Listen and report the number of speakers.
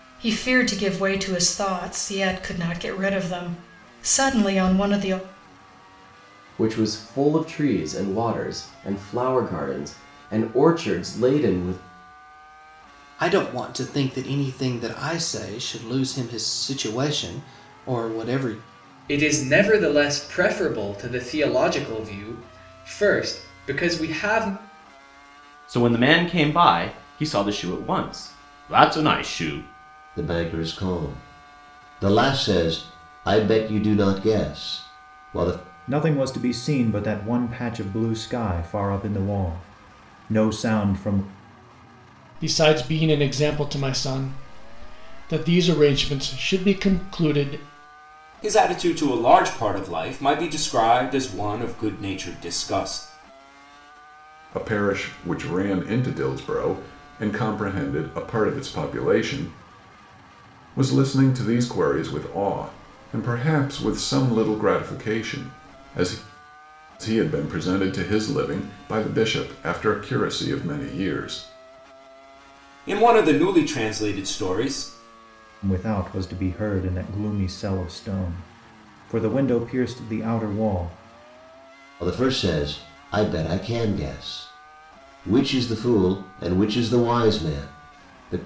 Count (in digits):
10